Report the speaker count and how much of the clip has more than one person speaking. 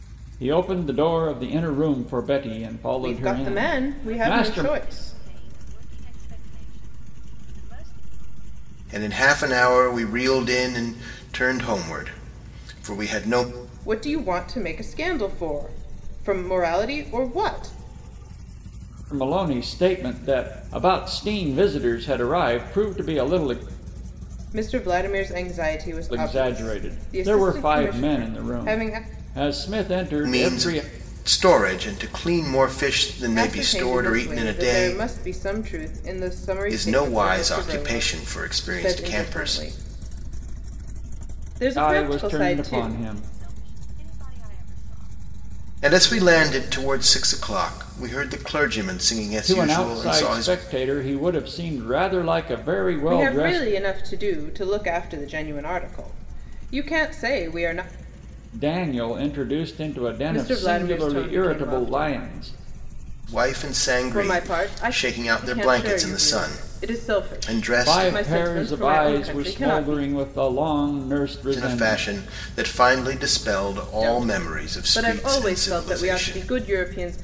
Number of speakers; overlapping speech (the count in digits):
4, about 34%